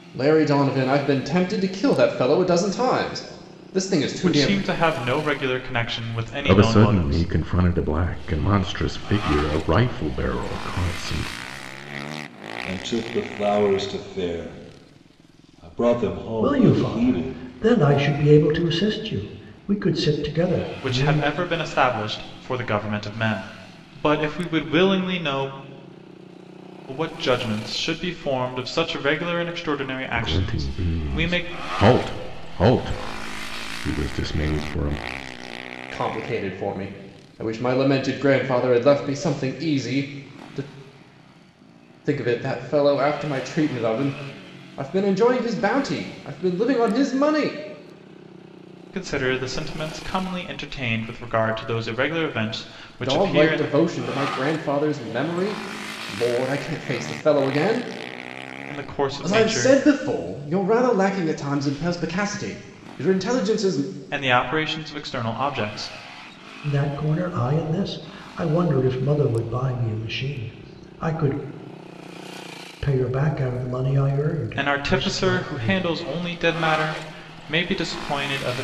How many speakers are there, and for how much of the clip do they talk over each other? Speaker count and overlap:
5, about 9%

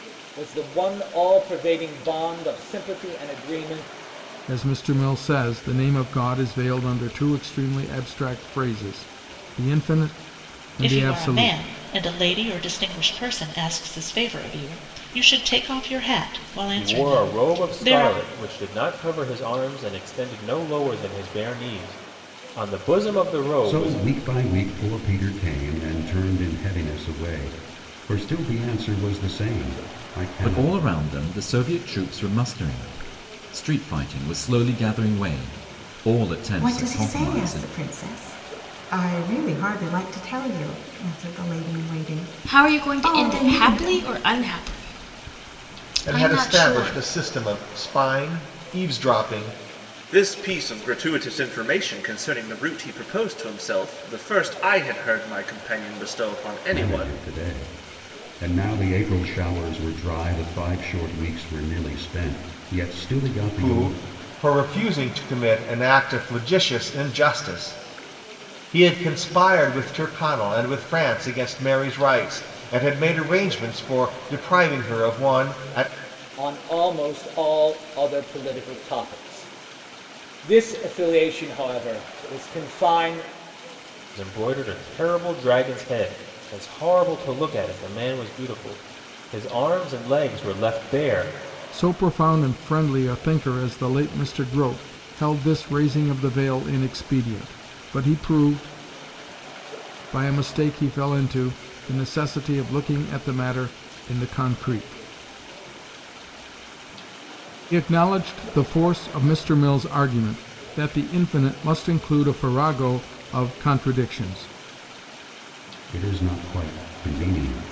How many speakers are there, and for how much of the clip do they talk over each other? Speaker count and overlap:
10, about 7%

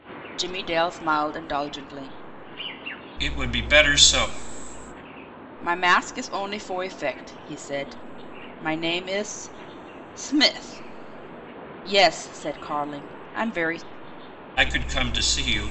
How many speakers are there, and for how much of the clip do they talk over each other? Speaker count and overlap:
2, no overlap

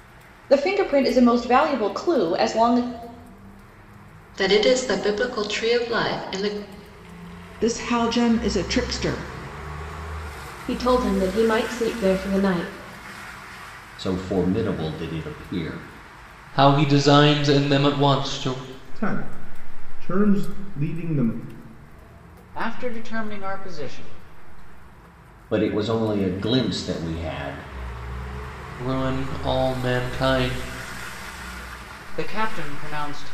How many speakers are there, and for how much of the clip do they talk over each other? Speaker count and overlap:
8, no overlap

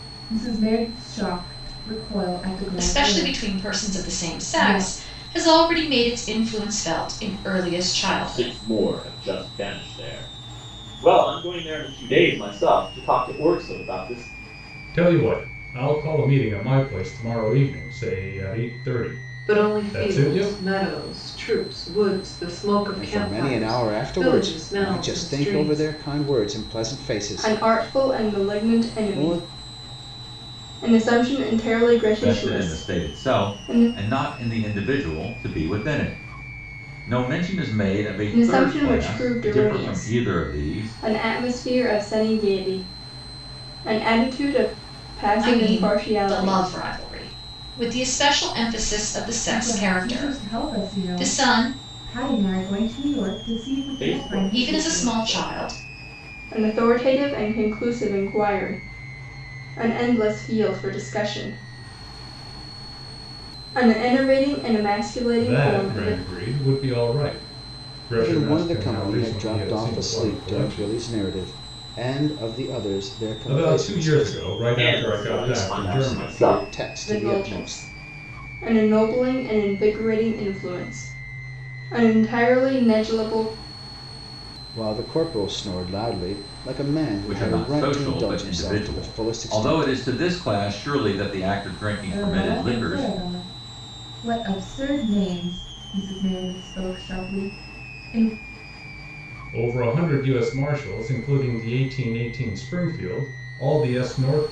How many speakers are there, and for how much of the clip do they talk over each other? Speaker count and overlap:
8, about 29%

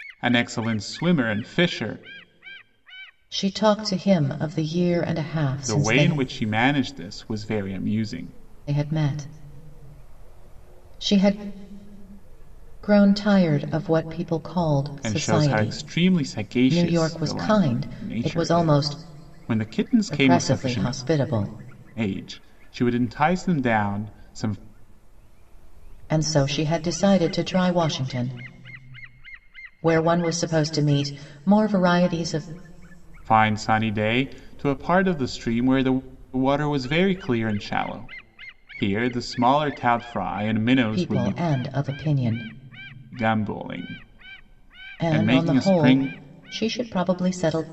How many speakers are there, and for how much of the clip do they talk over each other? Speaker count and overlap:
2, about 12%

